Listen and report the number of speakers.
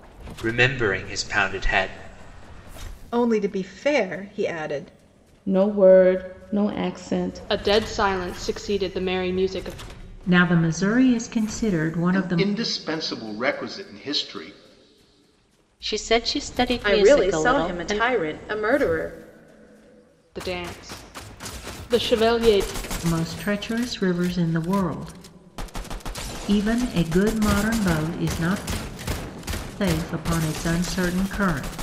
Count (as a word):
eight